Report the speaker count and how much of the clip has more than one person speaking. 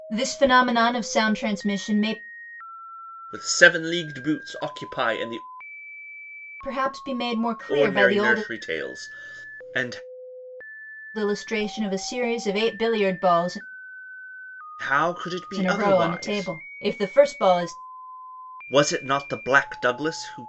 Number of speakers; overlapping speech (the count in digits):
2, about 9%